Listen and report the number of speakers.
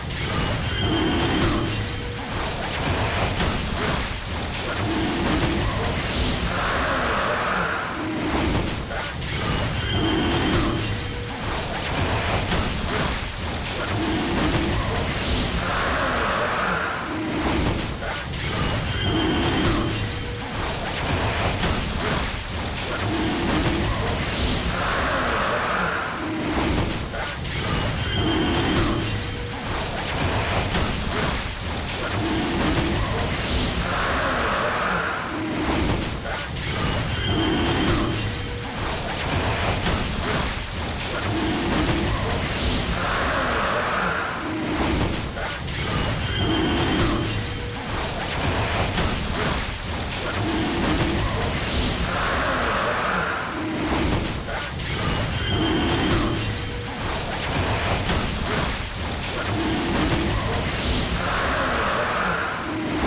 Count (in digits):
0